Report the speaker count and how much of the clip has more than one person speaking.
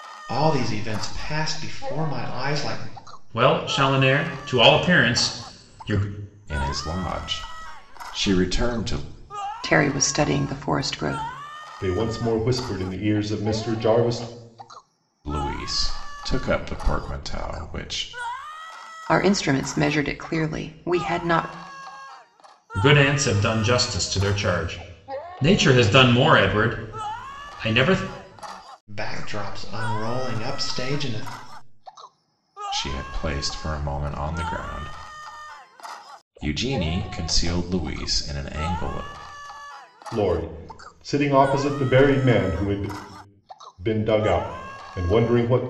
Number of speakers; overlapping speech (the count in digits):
5, no overlap